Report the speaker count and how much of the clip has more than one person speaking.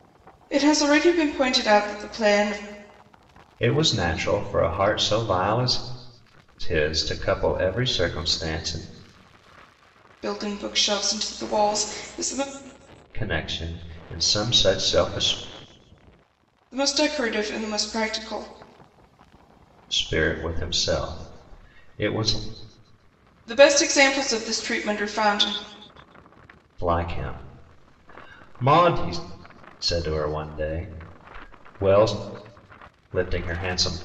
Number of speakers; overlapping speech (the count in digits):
2, no overlap